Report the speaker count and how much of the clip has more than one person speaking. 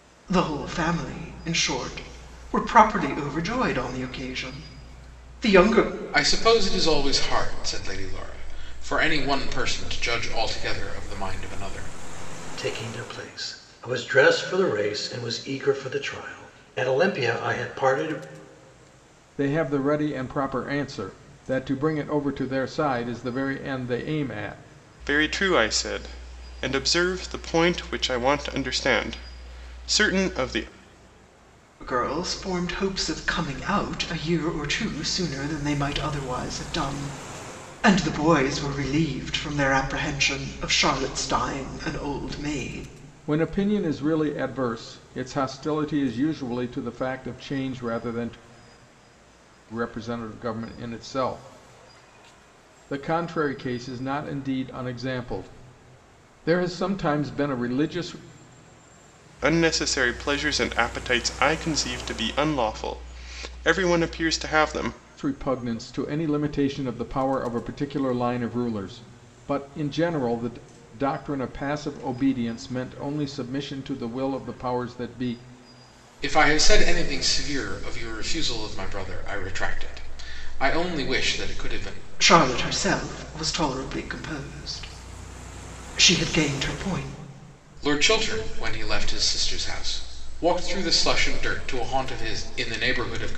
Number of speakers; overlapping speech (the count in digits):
5, no overlap